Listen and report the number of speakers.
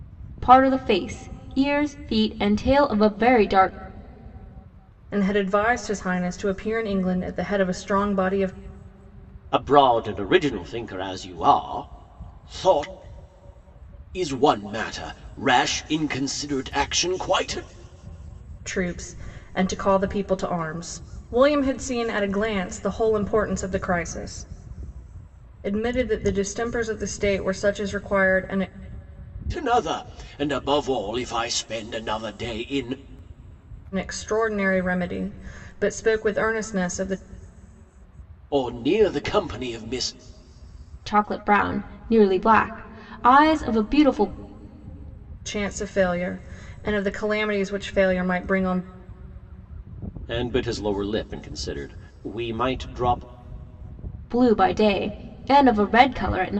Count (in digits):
3